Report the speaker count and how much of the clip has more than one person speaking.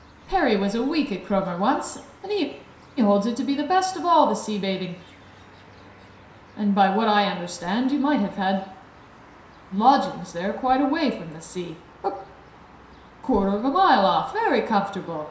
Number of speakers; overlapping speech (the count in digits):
1, no overlap